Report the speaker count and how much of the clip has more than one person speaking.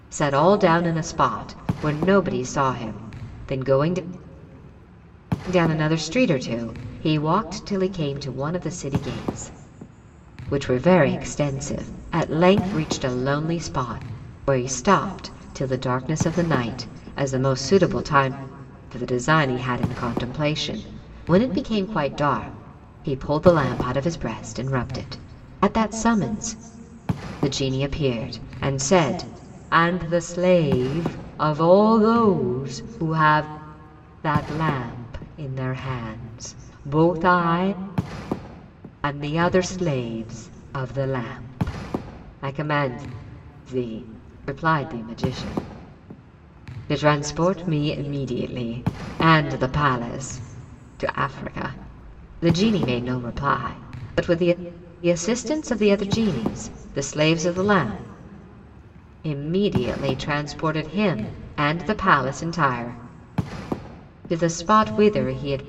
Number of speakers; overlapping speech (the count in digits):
1, no overlap